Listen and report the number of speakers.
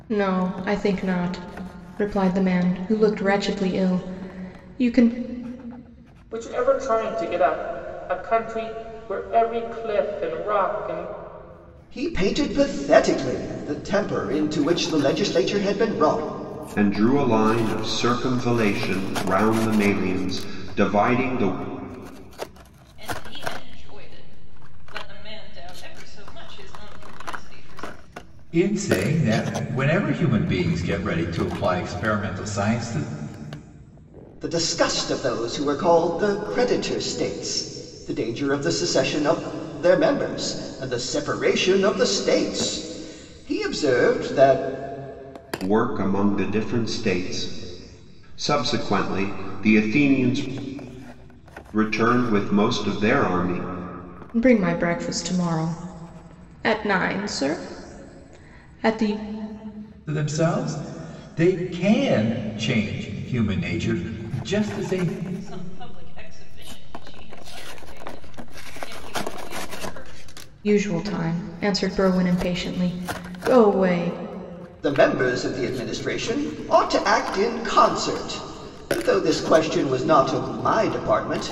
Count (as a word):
six